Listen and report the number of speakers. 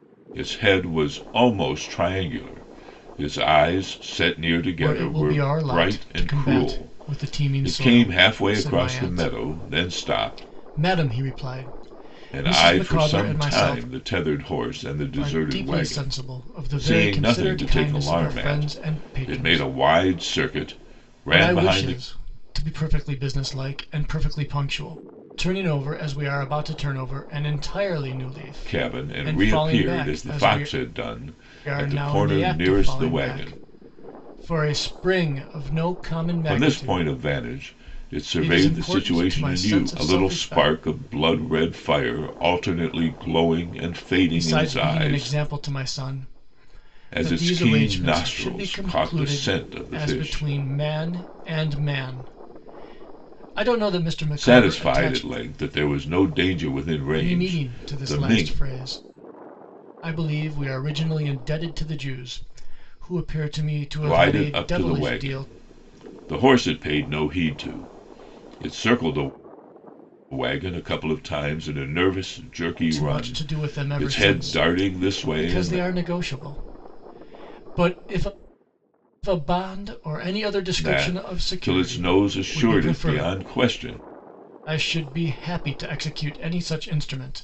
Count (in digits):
2